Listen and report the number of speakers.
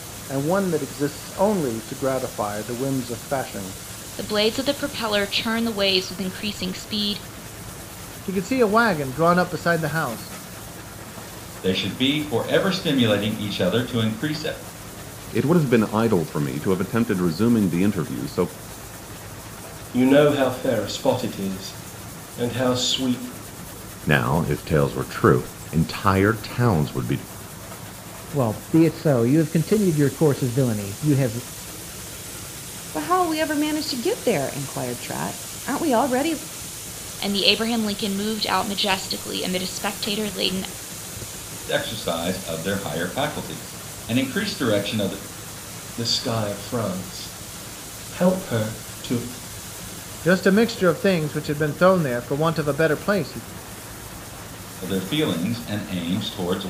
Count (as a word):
nine